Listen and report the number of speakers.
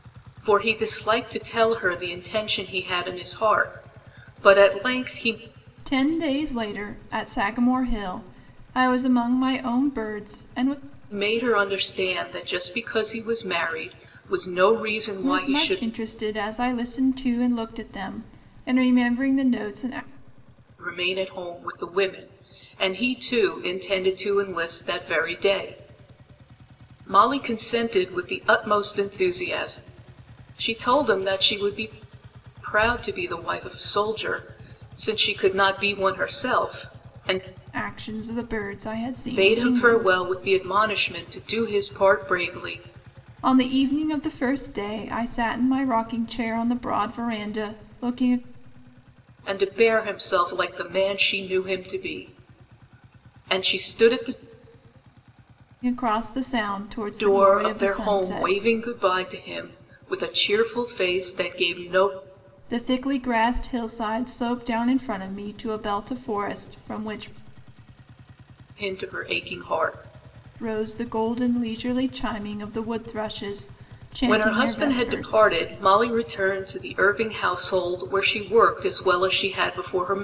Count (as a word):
two